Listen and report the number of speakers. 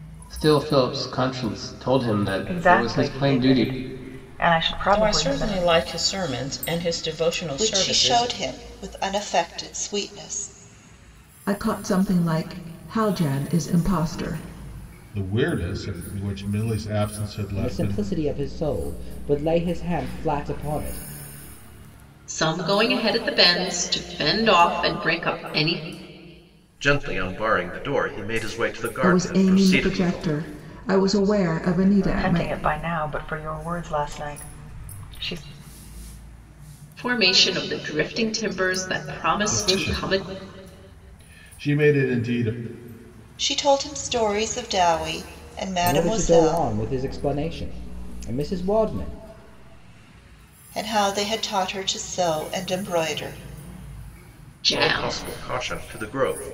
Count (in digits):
9